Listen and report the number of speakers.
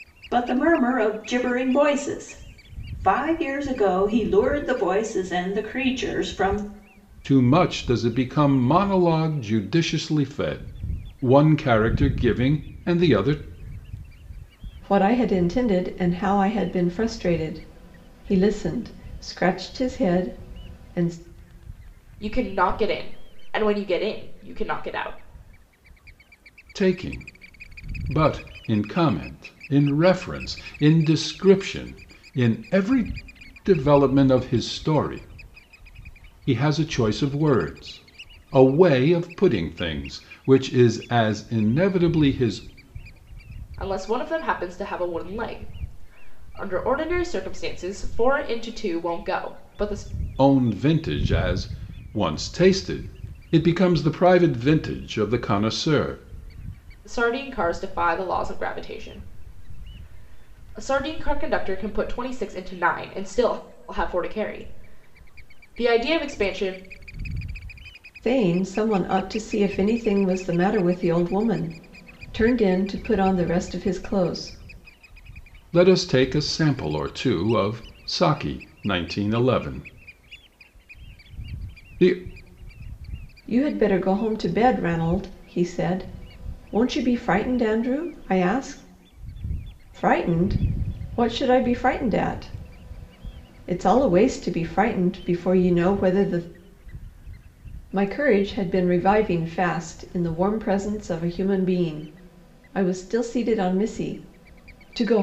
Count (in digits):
4